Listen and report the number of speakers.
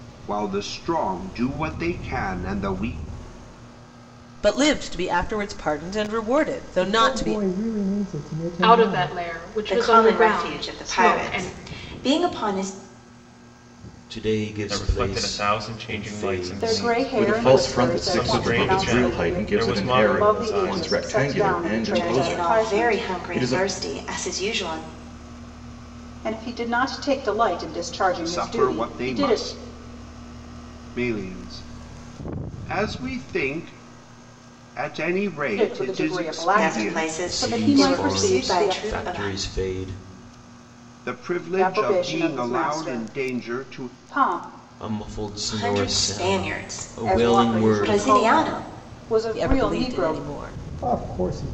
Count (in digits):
9